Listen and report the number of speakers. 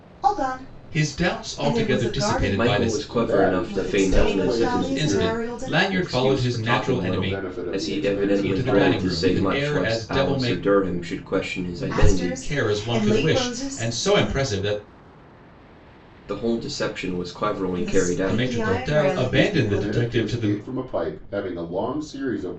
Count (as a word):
four